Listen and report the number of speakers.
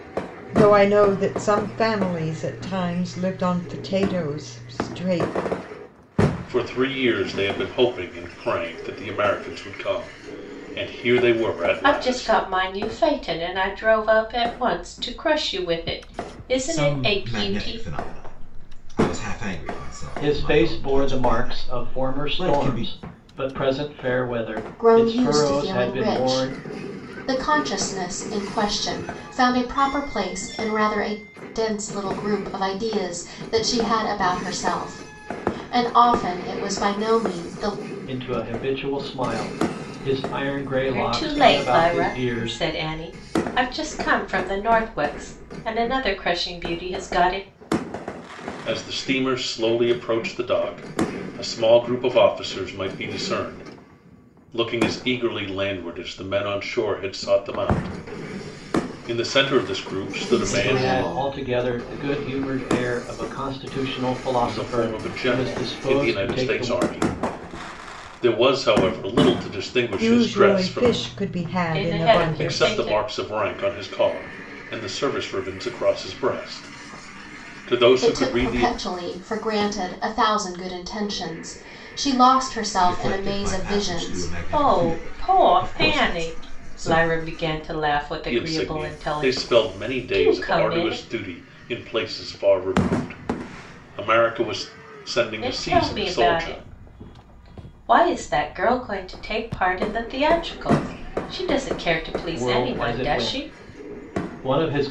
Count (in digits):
6